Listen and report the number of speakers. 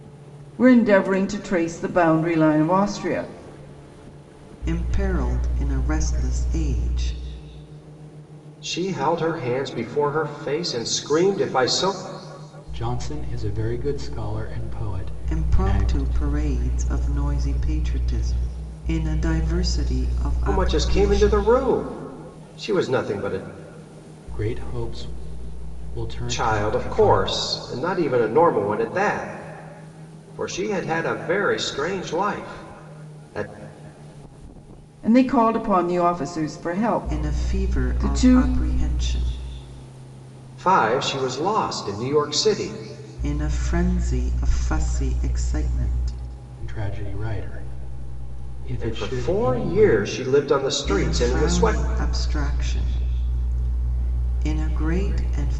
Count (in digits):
4